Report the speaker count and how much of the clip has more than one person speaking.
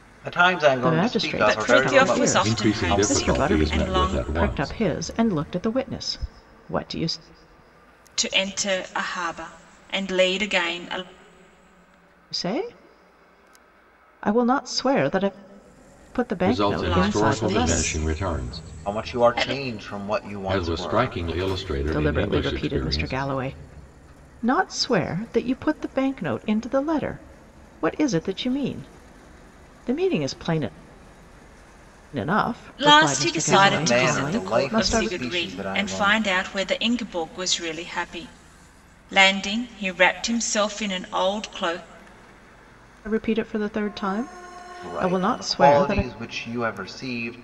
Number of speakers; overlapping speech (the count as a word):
four, about 29%